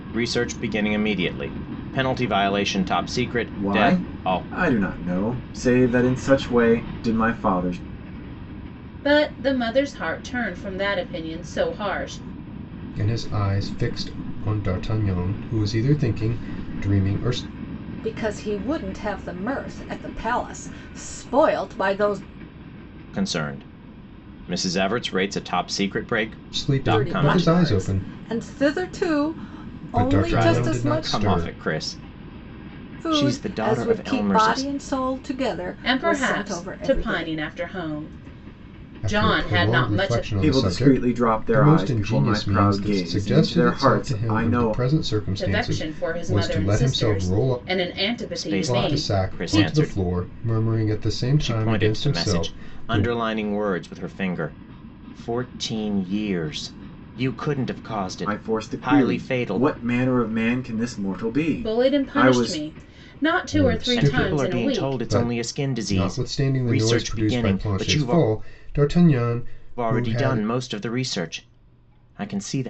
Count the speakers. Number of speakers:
5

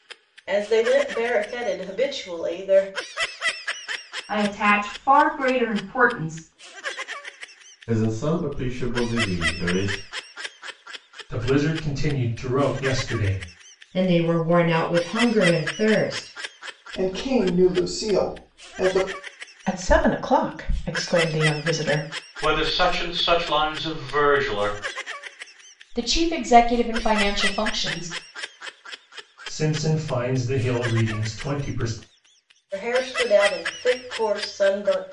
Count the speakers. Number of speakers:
9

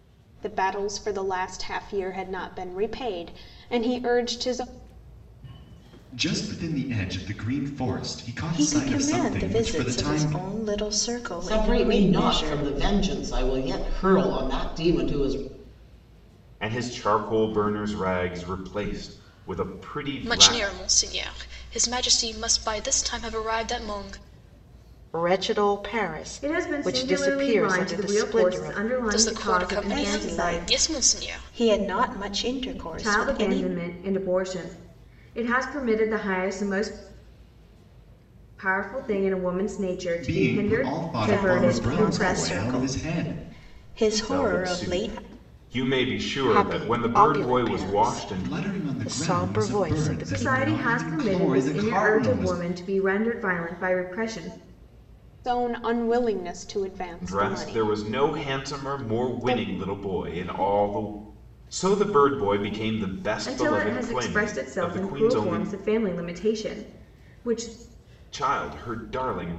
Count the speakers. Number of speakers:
8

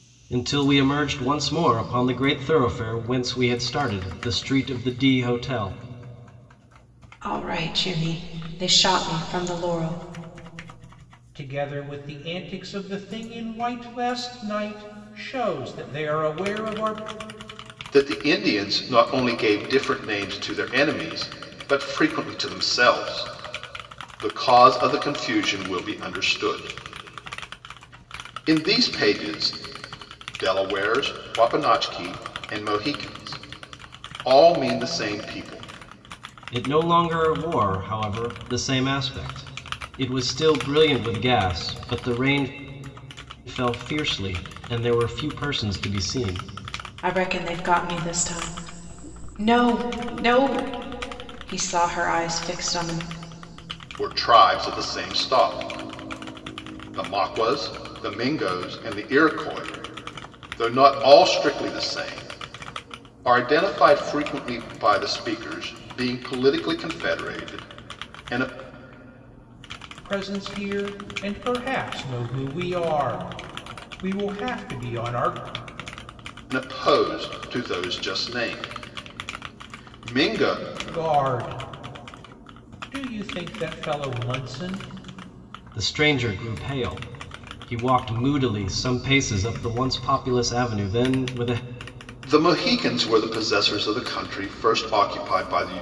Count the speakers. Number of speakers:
4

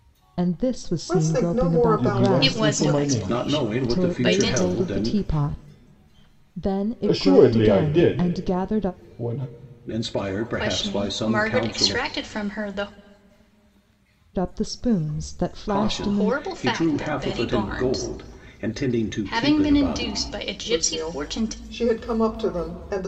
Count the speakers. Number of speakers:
5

